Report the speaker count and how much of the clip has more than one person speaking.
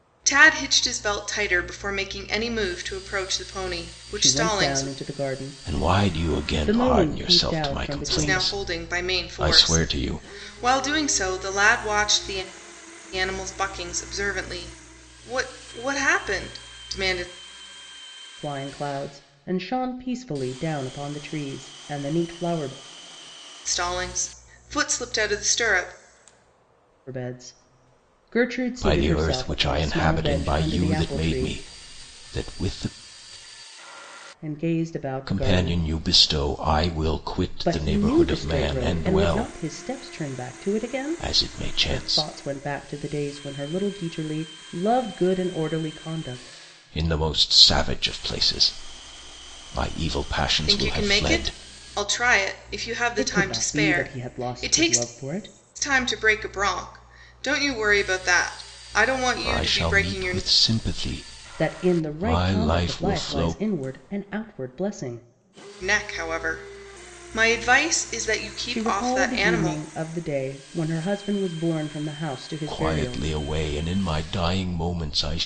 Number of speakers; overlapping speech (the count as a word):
three, about 26%